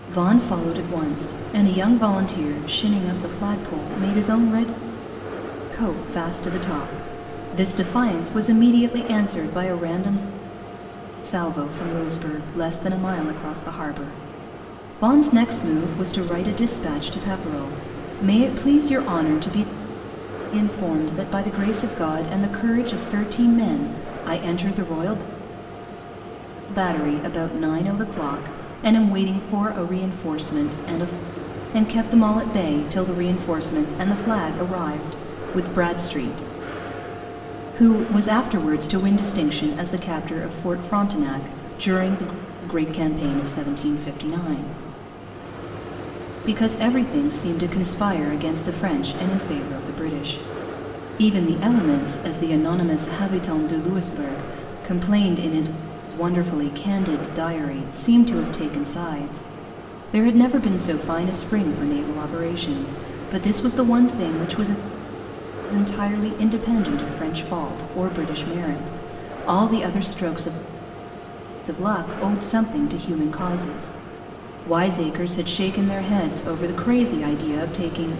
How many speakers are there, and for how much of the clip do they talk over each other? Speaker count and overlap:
1, no overlap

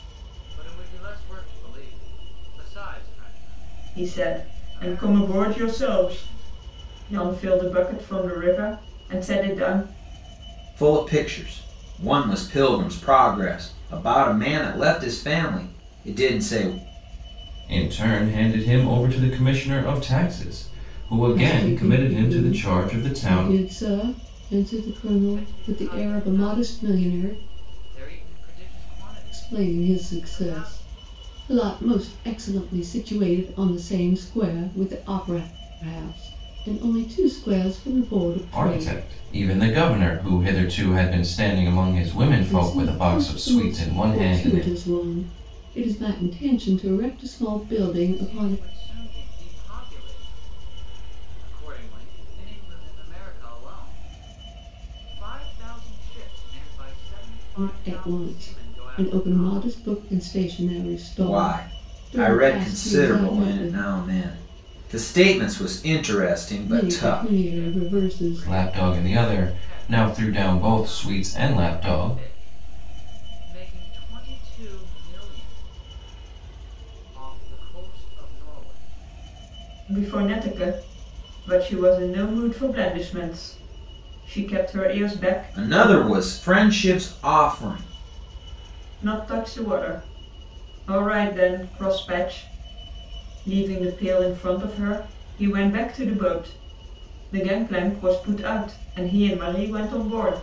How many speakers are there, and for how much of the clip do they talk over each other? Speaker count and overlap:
5, about 23%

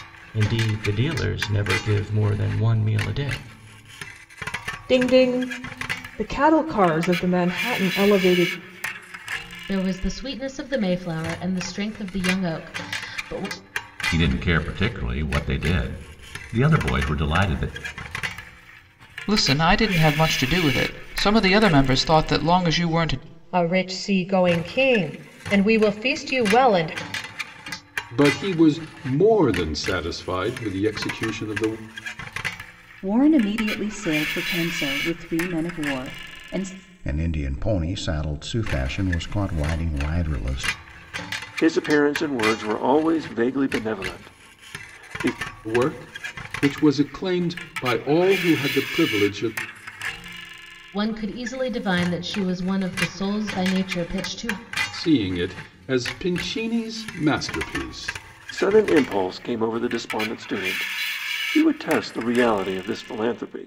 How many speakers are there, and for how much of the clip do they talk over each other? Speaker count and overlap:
10, no overlap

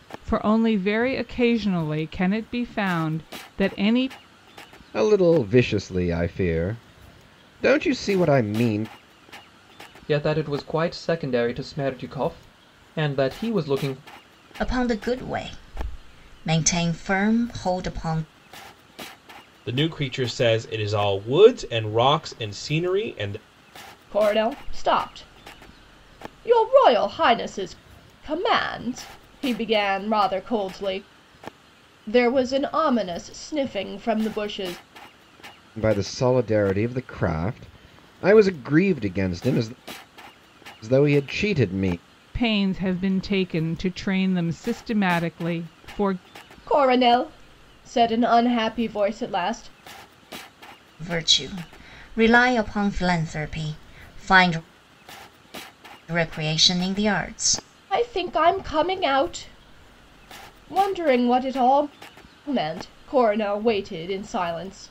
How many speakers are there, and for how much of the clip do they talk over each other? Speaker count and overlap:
6, no overlap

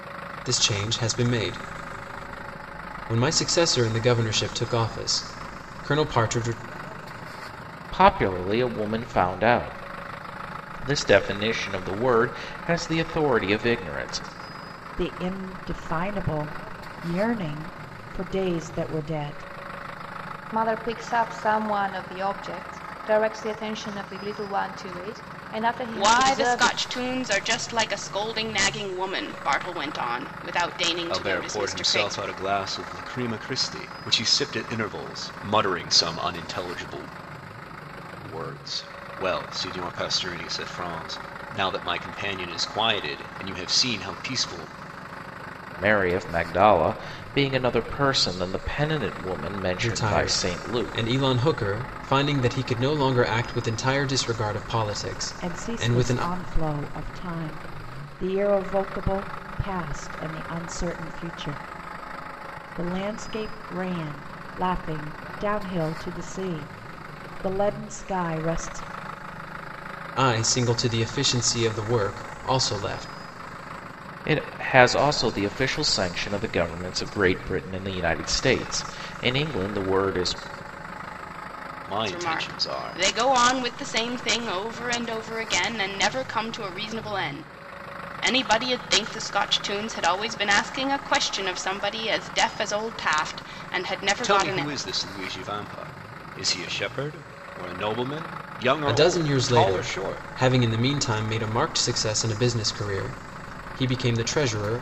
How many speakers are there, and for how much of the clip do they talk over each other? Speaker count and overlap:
6, about 7%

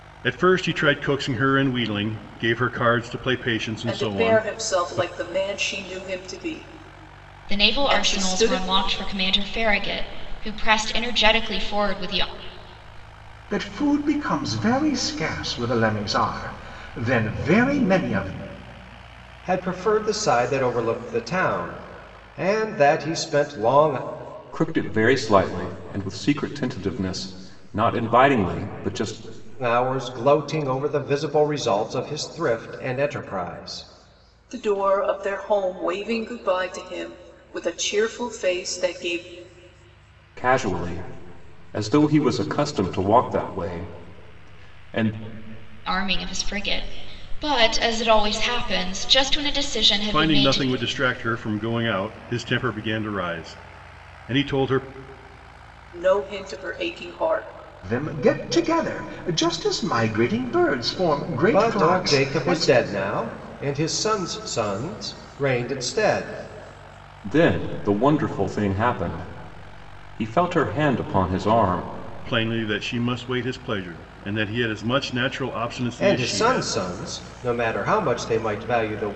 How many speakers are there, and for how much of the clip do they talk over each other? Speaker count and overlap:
6, about 7%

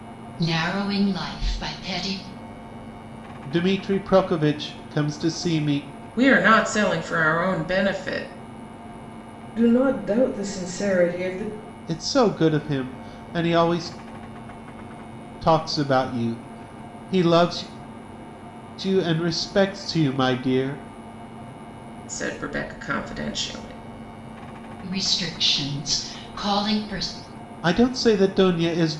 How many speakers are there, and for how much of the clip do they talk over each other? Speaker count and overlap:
4, no overlap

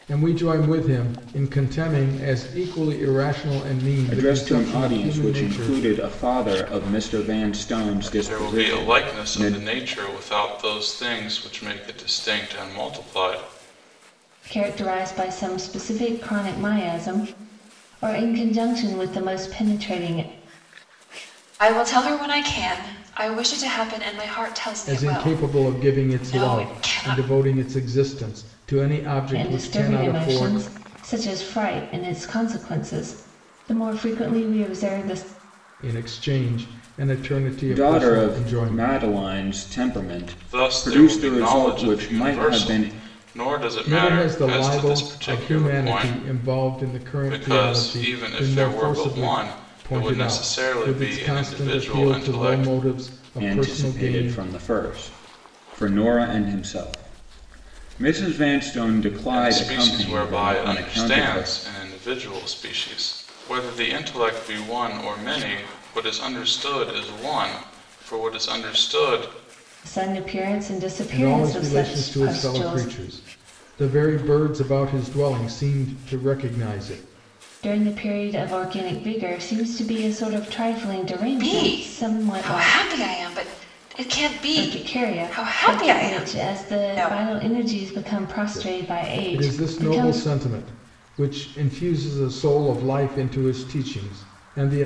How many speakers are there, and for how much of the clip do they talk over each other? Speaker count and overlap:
5, about 31%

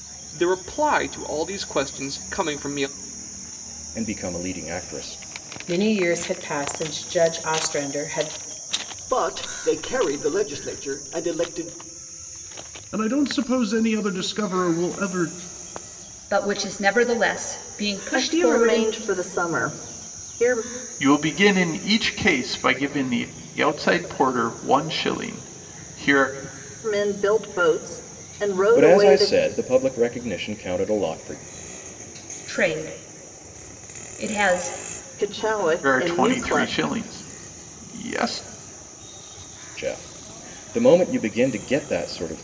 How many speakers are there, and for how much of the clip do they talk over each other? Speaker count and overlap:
8, about 6%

